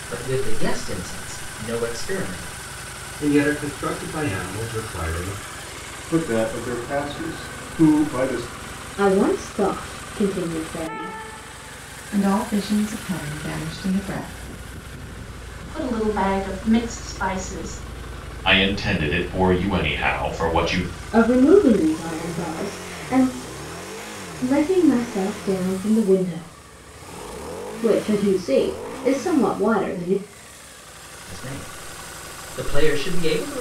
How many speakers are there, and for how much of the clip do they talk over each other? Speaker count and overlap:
7, no overlap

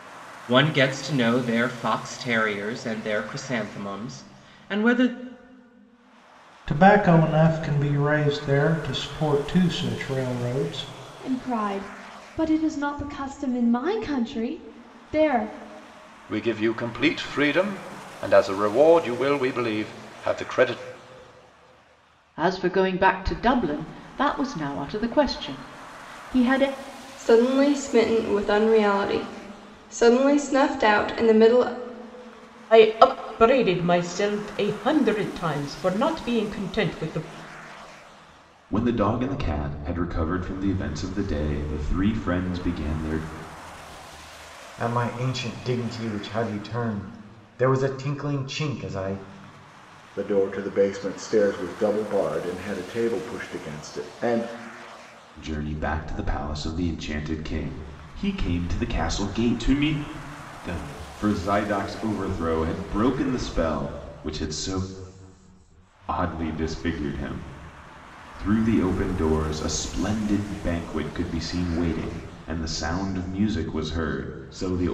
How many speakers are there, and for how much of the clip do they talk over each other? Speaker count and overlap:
10, no overlap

